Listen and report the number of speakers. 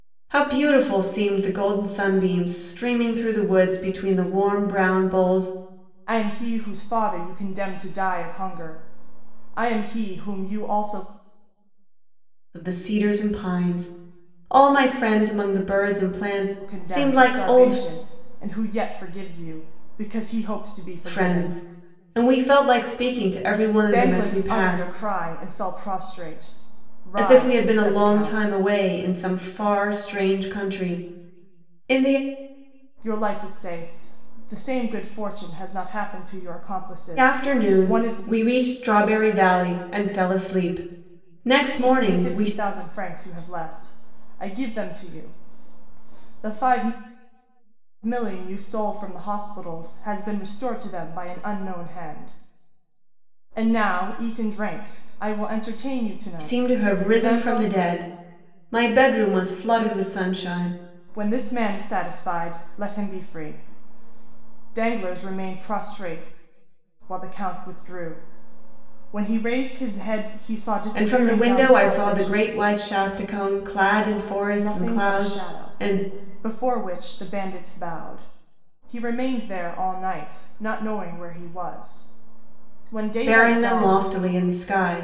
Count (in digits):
2